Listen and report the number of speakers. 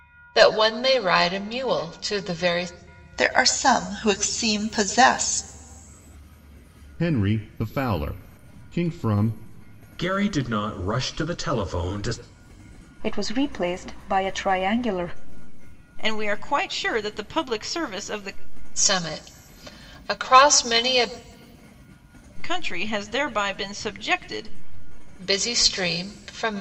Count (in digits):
6